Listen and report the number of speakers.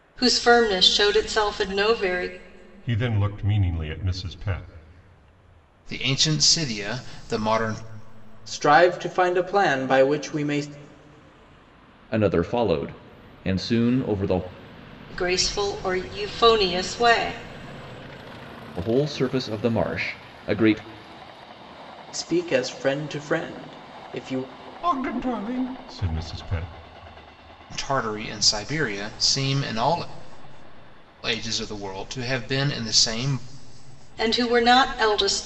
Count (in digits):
5